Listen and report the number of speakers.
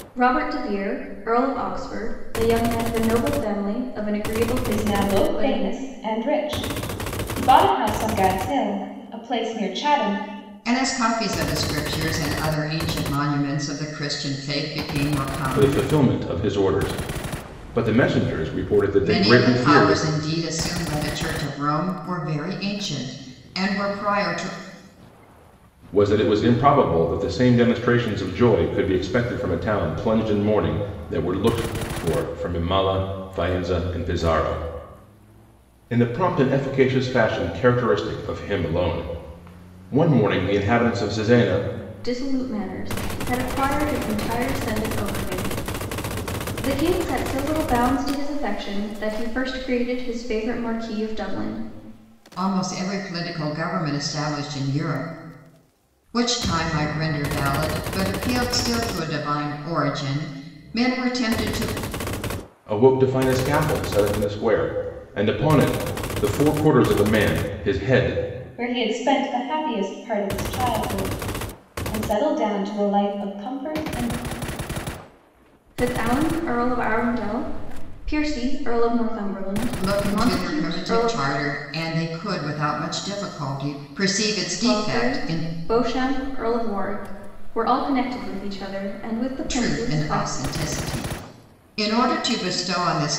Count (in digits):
4